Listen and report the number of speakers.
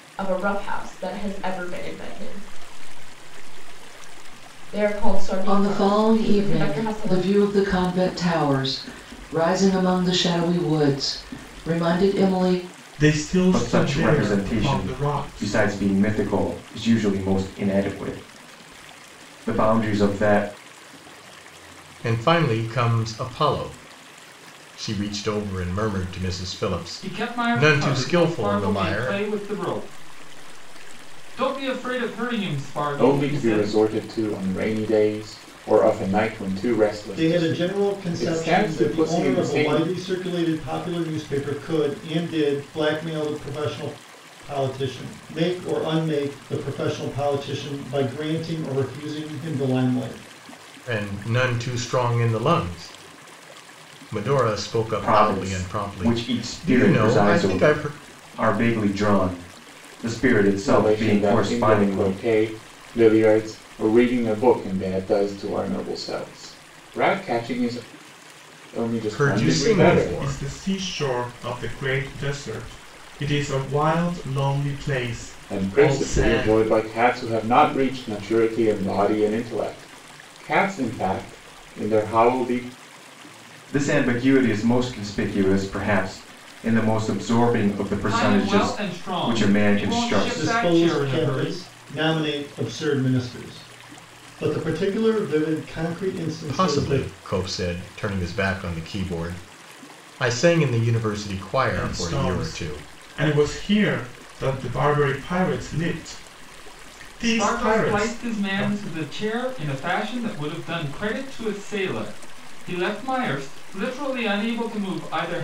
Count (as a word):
eight